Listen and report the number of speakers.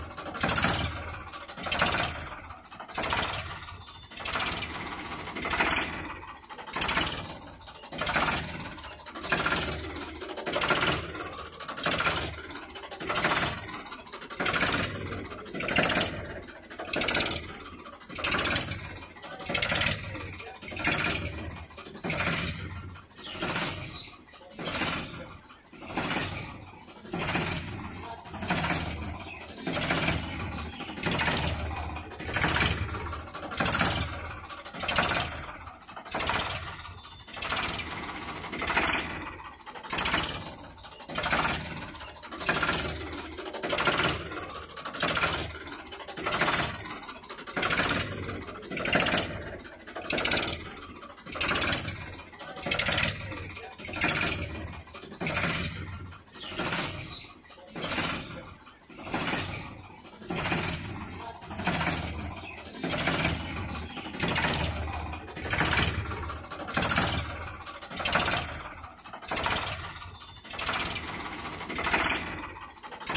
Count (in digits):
0